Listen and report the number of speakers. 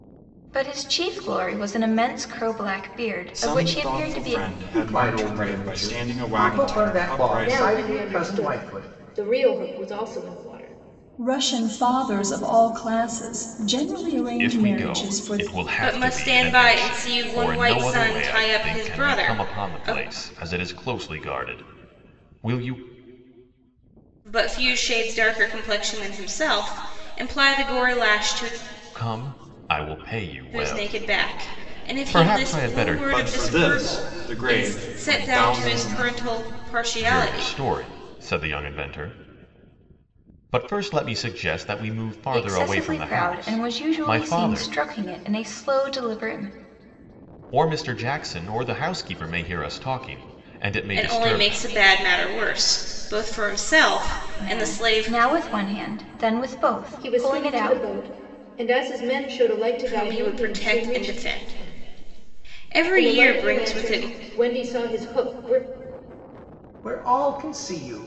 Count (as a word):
seven